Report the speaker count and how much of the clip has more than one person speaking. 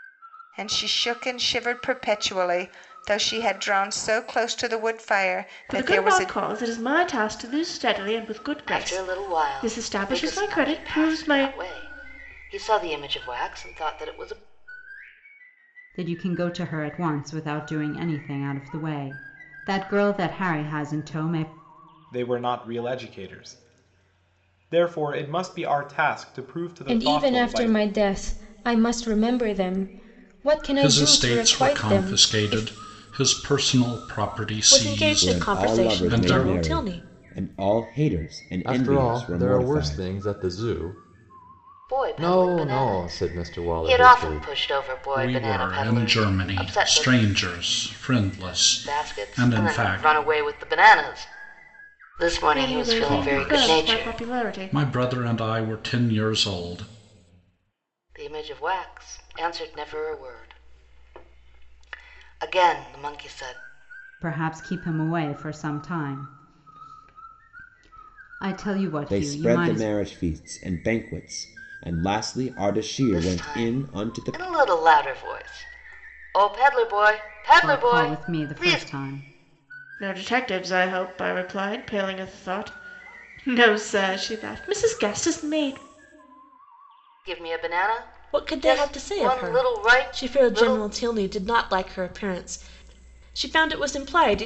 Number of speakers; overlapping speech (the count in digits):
10, about 26%